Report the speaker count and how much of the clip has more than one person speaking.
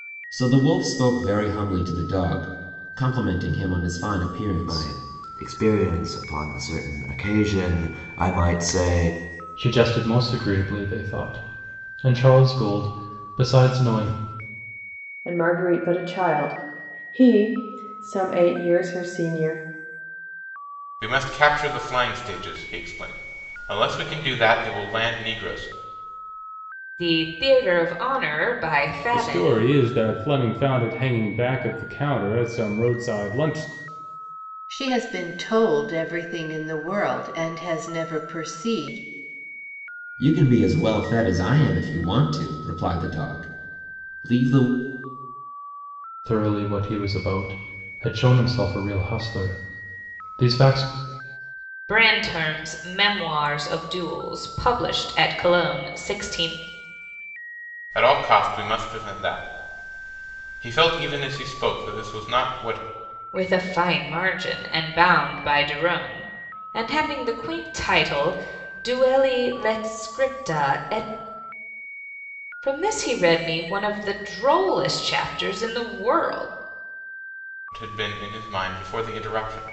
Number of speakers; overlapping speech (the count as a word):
eight, about 1%